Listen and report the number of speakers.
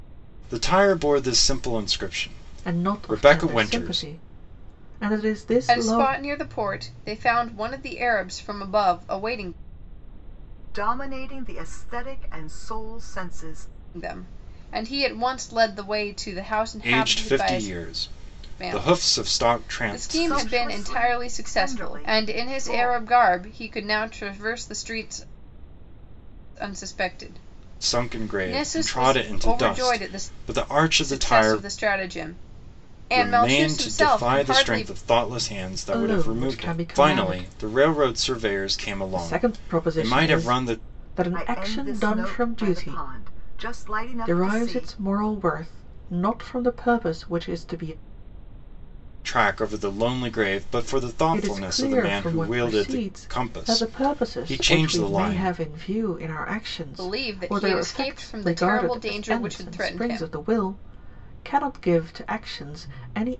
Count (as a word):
four